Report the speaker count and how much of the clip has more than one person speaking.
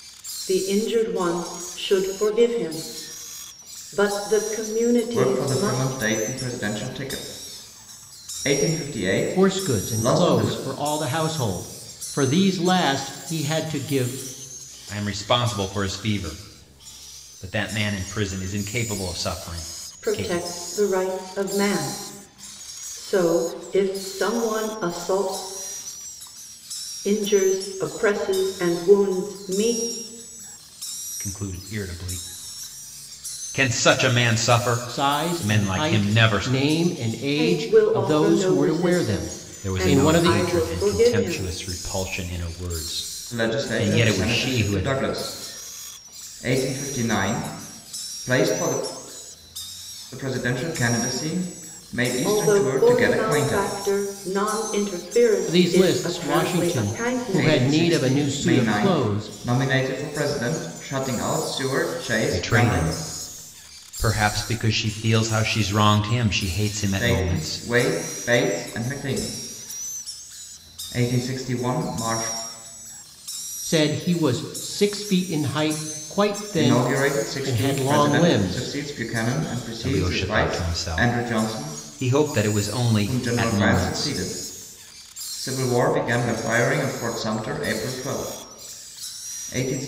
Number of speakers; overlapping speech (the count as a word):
four, about 25%